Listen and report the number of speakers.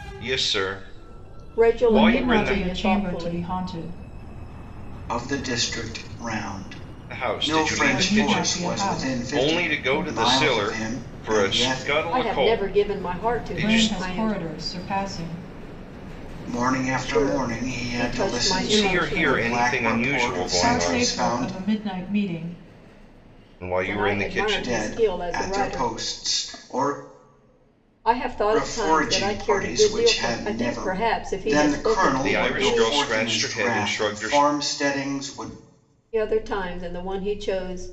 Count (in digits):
4